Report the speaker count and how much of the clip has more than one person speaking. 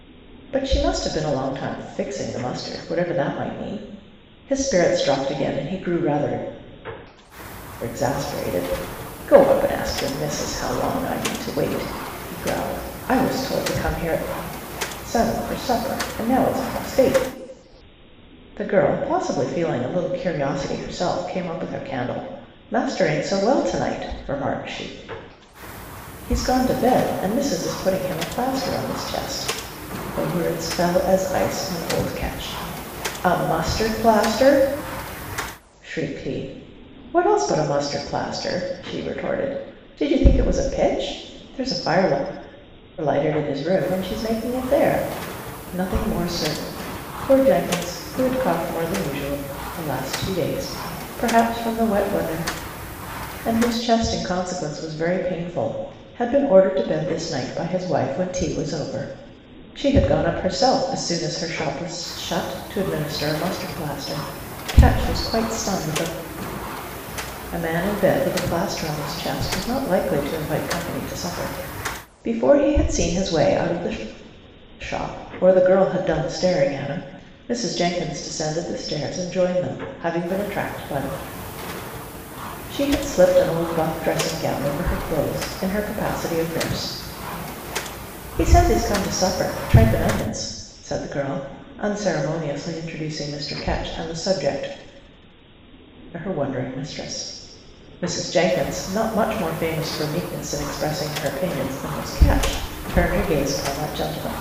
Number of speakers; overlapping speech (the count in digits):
1, no overlap